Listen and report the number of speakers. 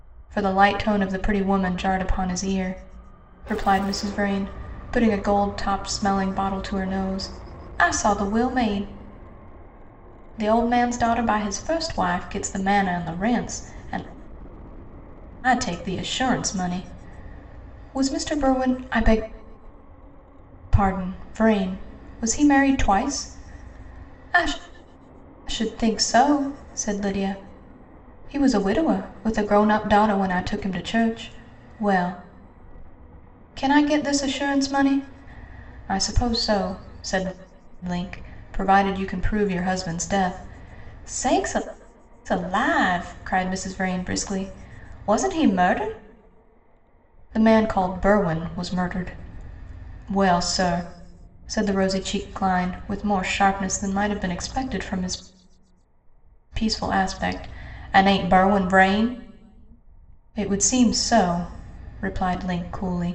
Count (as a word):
one